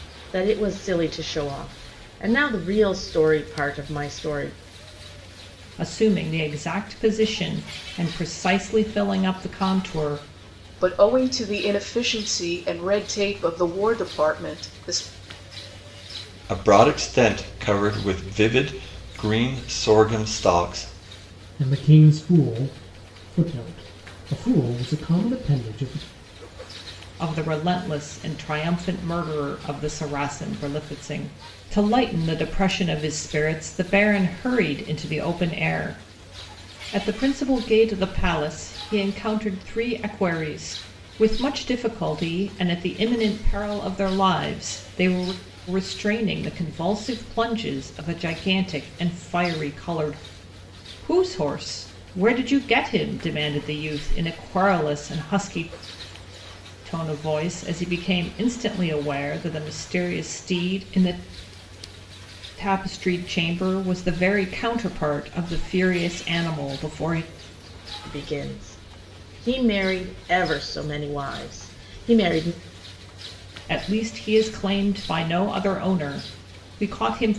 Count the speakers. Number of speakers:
5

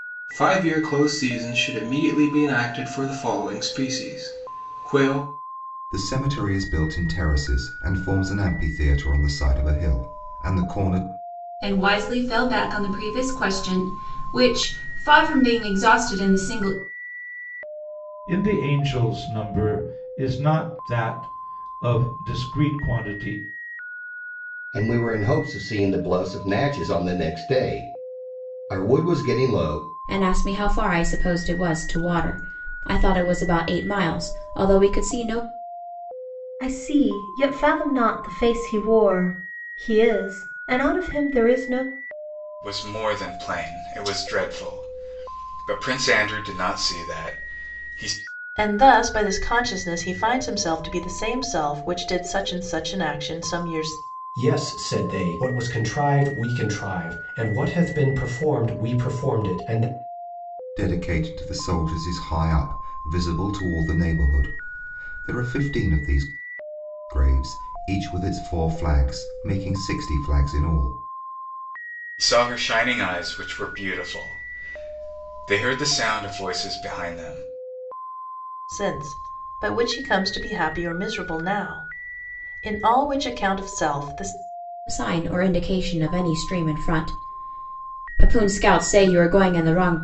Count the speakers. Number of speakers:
10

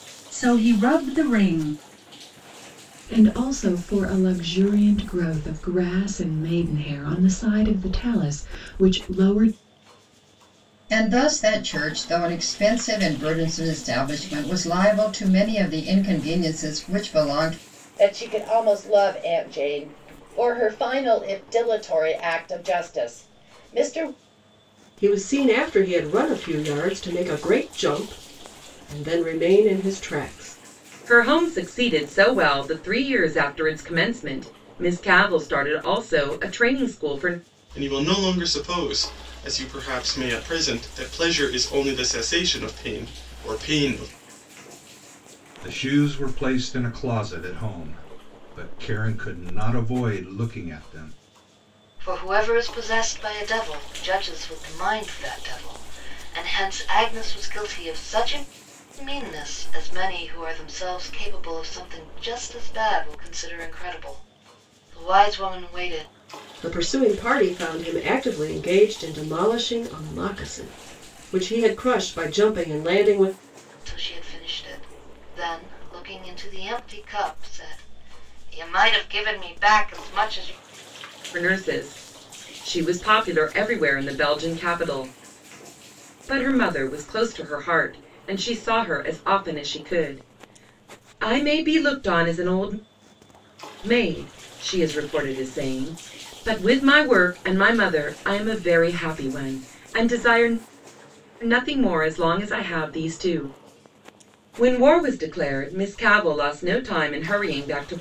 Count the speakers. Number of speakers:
9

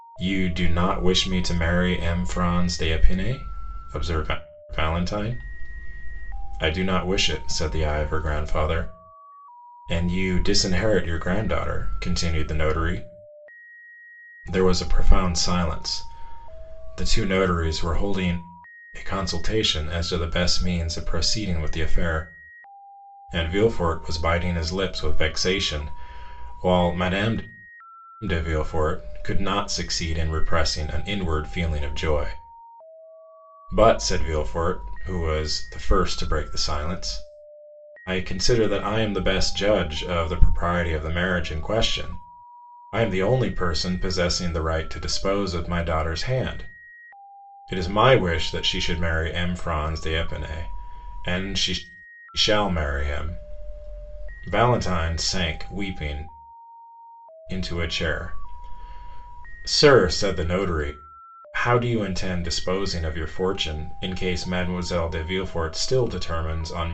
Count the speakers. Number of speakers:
1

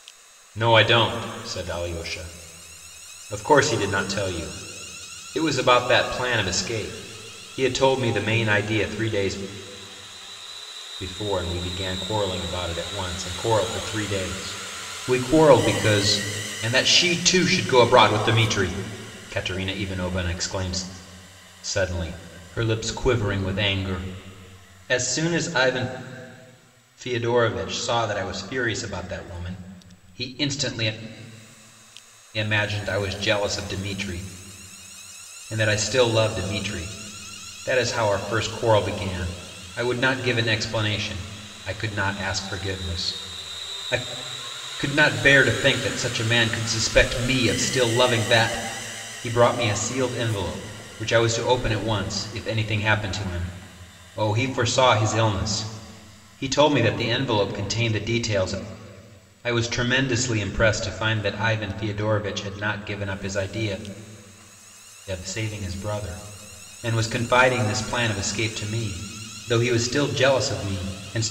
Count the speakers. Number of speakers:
1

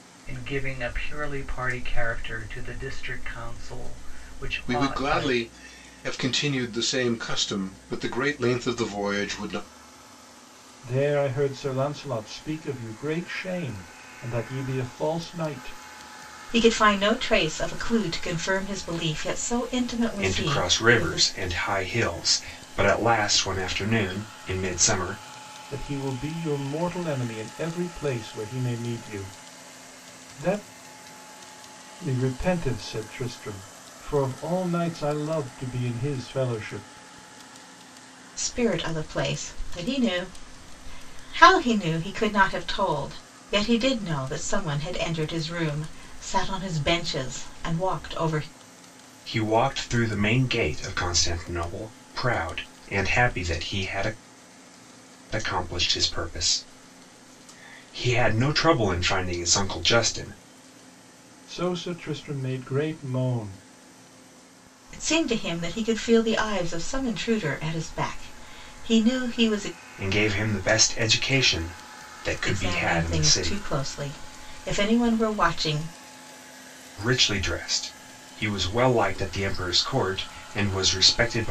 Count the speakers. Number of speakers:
5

